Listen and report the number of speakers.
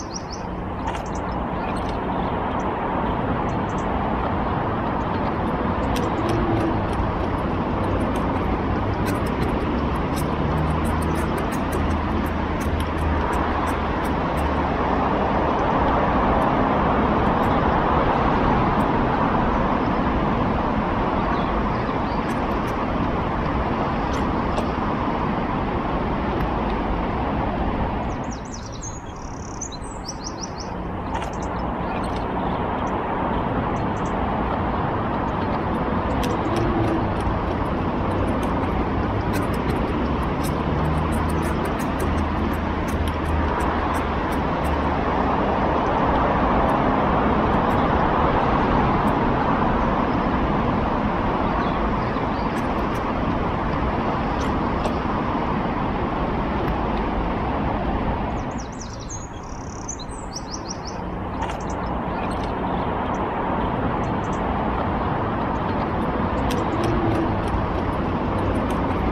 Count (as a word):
zero